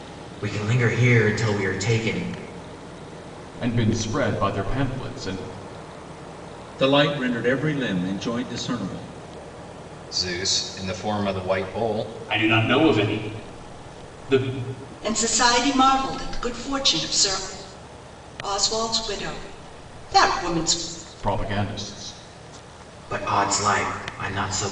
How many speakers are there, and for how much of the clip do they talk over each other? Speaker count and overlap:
6, no overlap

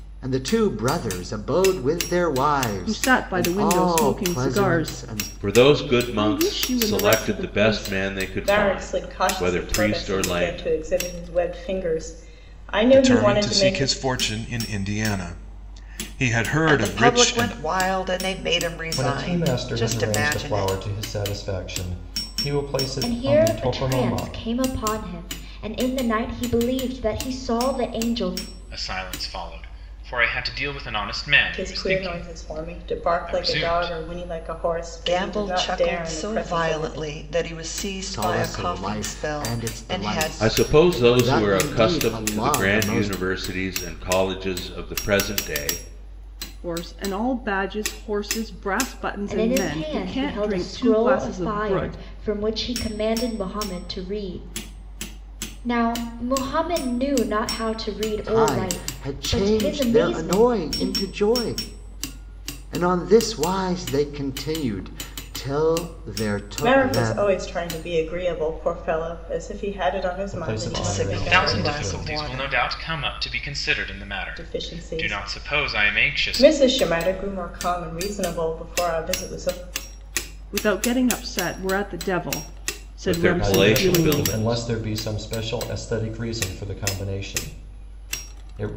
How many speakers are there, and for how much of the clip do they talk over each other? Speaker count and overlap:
9, about 39%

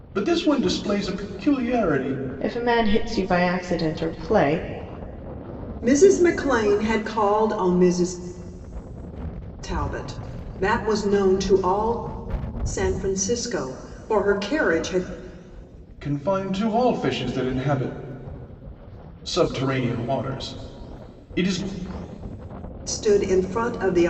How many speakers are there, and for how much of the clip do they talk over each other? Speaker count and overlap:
3, no overlap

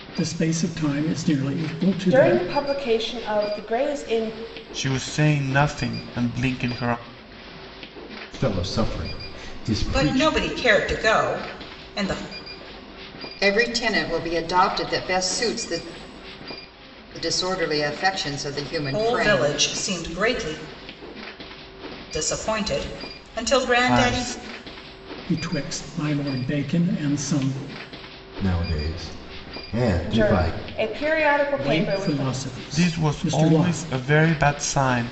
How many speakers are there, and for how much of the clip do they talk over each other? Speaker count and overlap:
6, about 13%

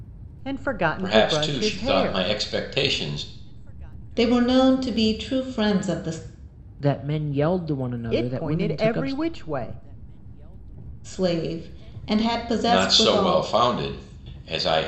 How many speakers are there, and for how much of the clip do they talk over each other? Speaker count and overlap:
4, about 21%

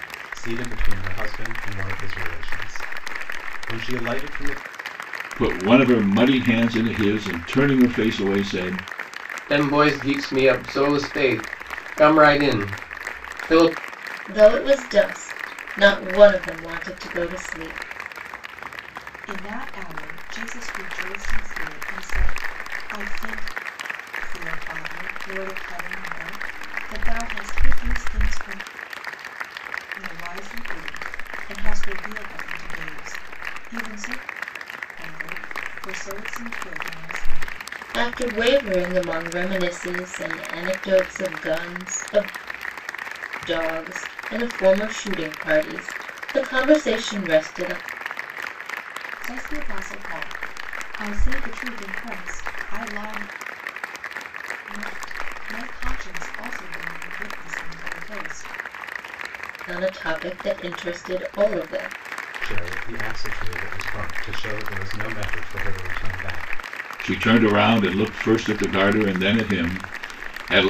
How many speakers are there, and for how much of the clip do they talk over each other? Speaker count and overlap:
5, no overlap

